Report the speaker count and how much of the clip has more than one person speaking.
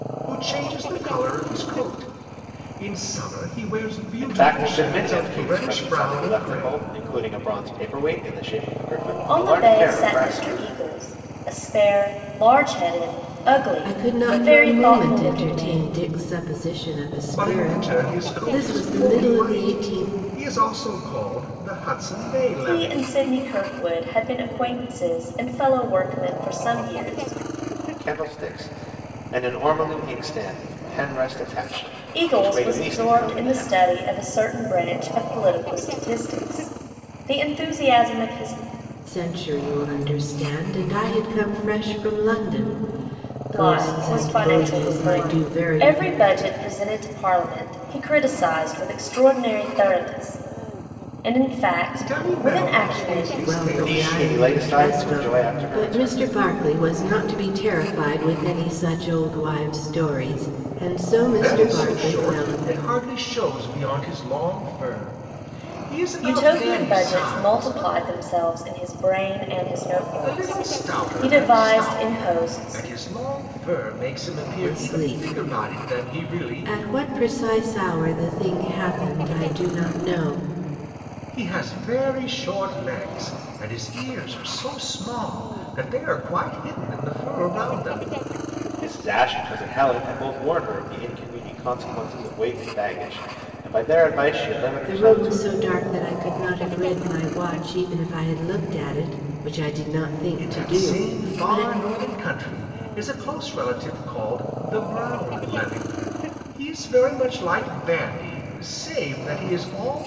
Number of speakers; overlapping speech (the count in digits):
4, about 25%